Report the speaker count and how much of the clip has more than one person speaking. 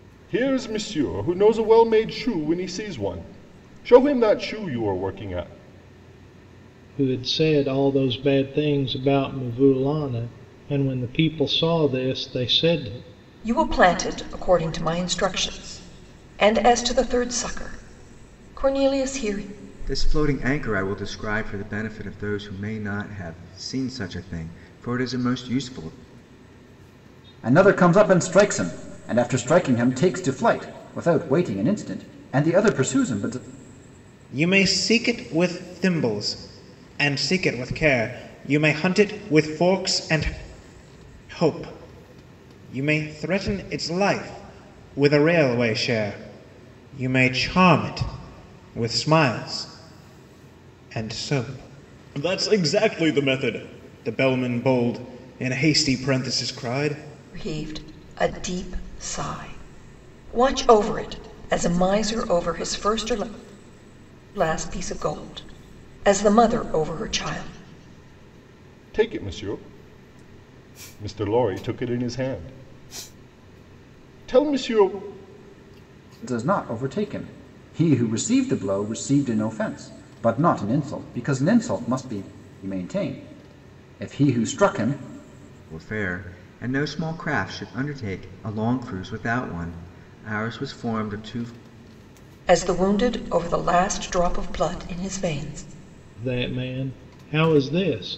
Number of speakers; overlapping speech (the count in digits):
6, no overlap